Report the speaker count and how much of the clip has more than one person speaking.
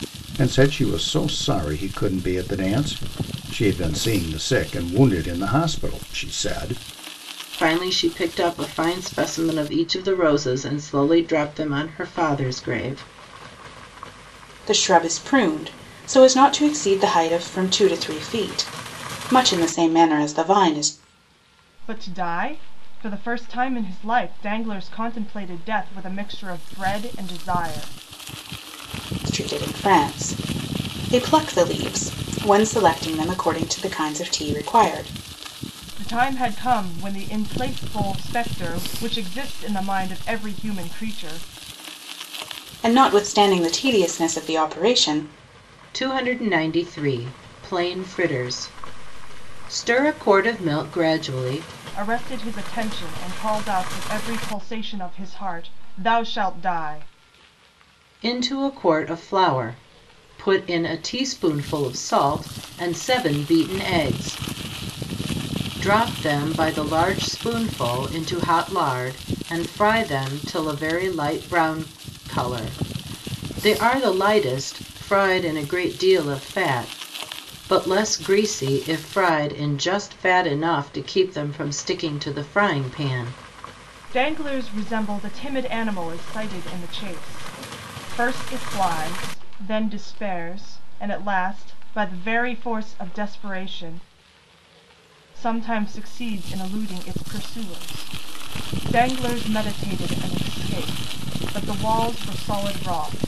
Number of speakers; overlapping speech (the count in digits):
4, no overlap